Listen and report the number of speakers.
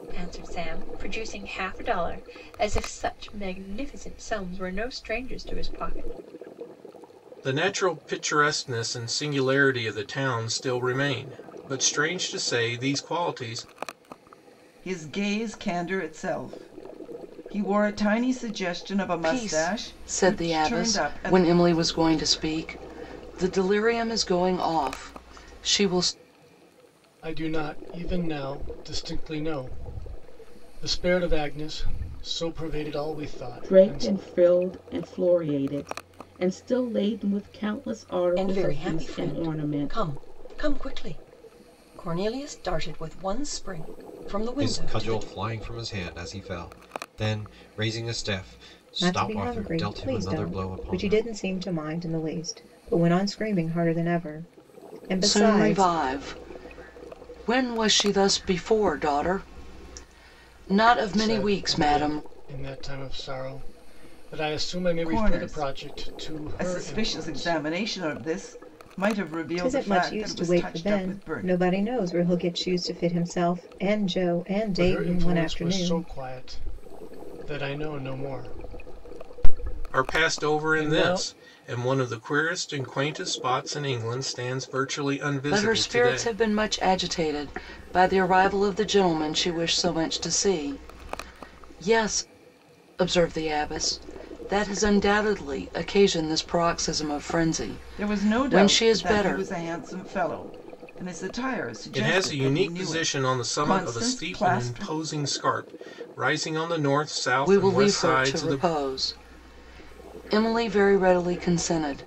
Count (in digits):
9